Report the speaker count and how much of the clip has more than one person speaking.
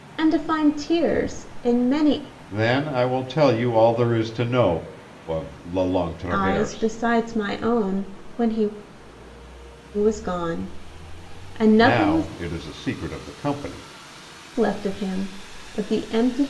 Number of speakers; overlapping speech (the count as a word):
two, about 7%